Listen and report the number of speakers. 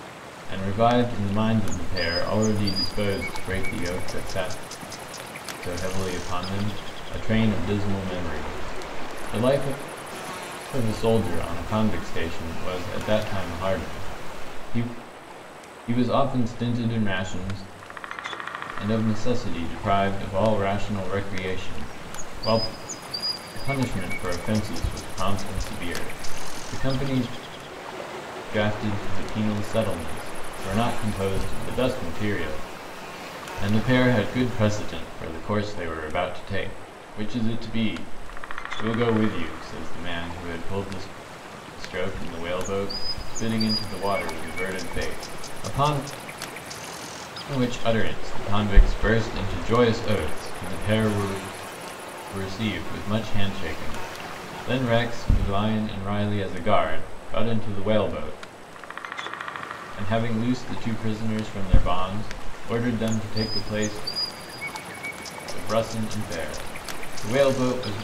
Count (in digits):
1